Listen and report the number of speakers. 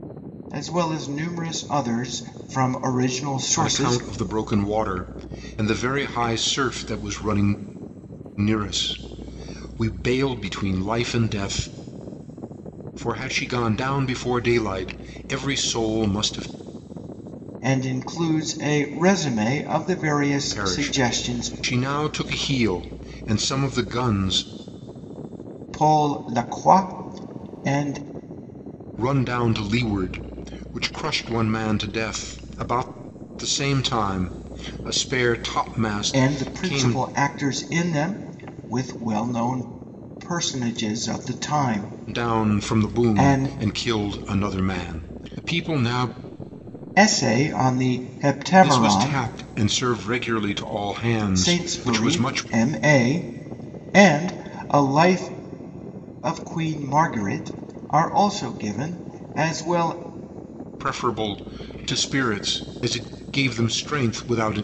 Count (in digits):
2